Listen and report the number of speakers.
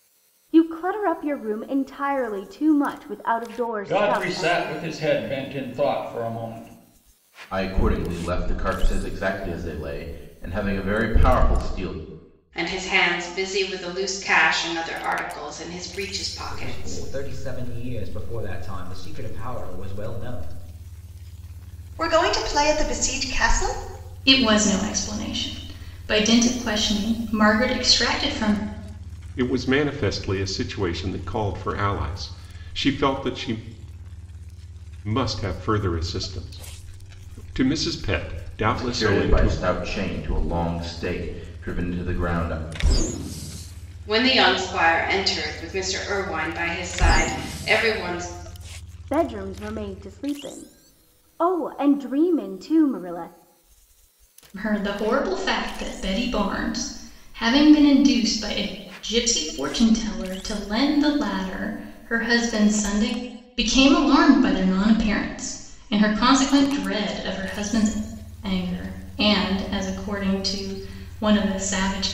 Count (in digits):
8